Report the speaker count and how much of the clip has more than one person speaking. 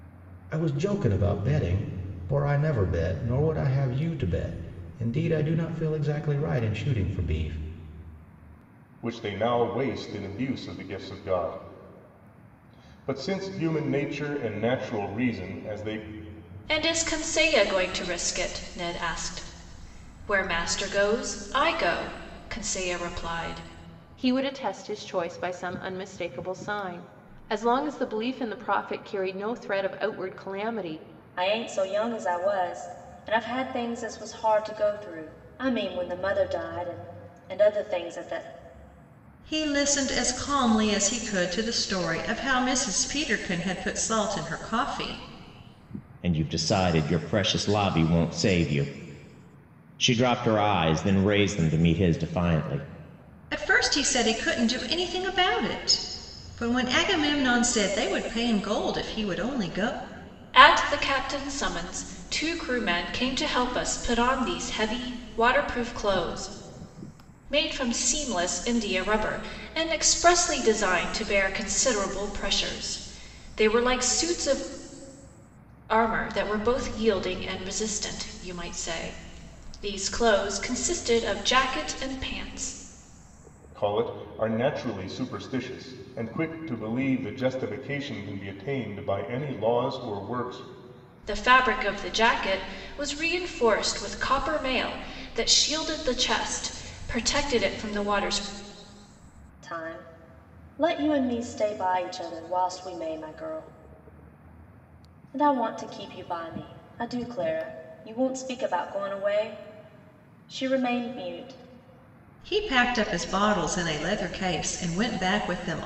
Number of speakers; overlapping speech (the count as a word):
seven, no overlap